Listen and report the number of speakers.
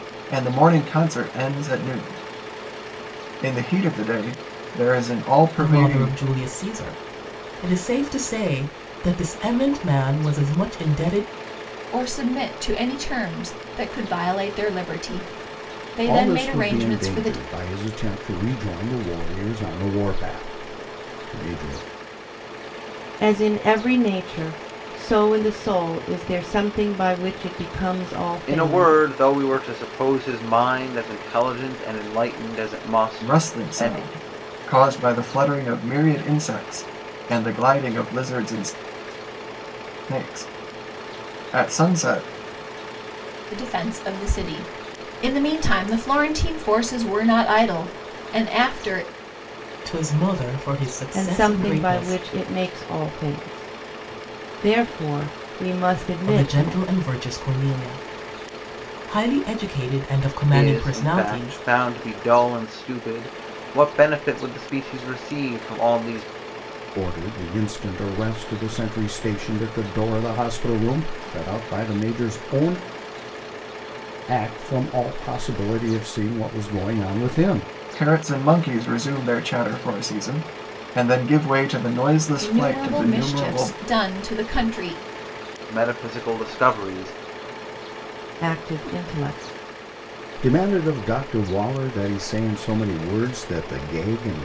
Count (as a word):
six